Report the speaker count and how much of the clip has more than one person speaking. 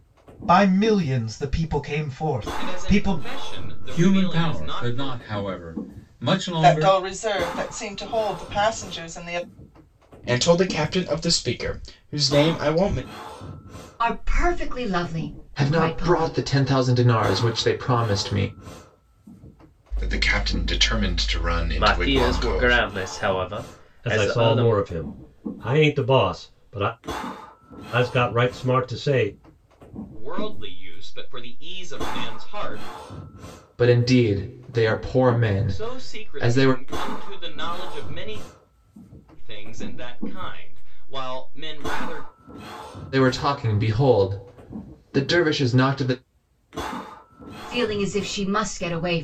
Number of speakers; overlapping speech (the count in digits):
10, about 13%